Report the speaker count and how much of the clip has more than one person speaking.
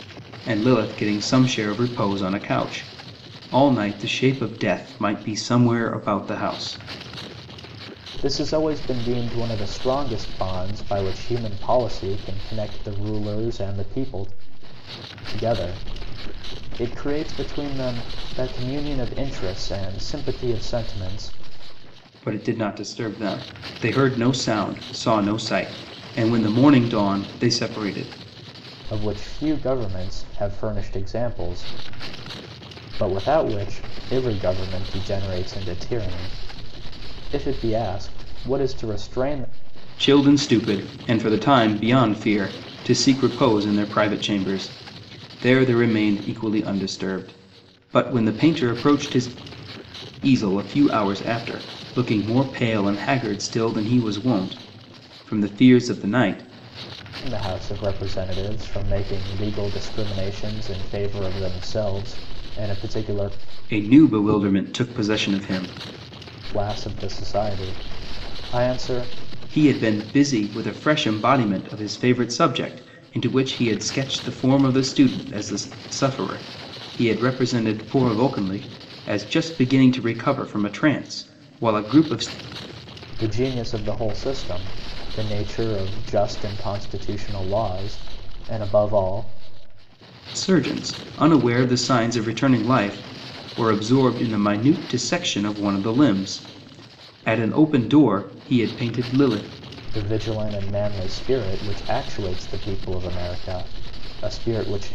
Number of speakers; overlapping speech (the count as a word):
two, no overlap